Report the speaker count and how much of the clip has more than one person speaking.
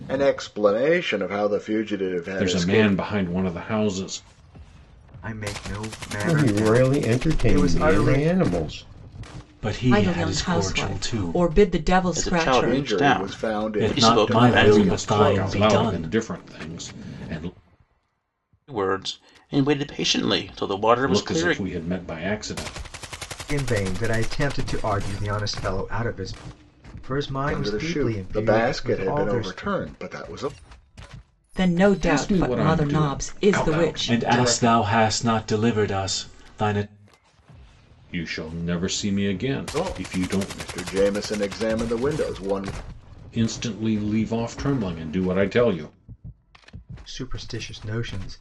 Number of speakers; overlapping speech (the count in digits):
7, about 30%